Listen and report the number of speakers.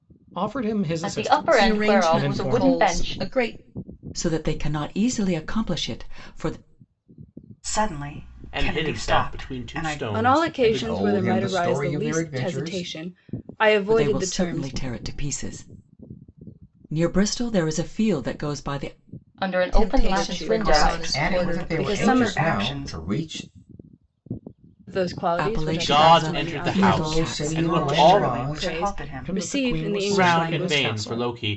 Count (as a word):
eight